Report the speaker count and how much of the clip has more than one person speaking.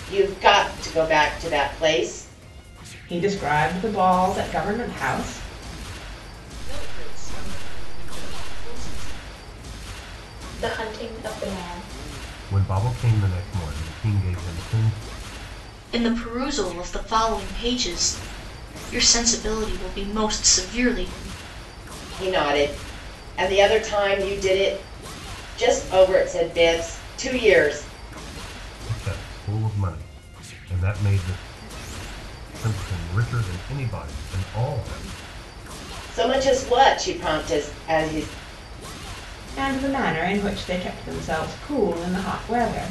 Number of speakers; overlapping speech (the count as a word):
six, no overlap